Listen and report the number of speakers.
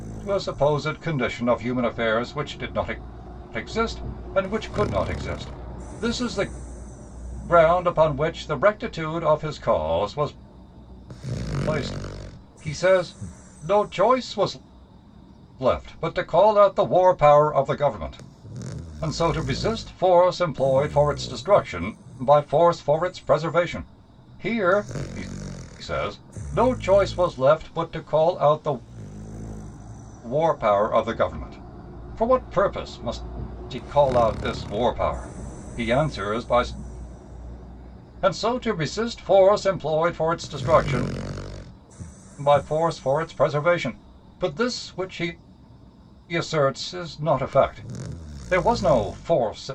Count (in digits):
1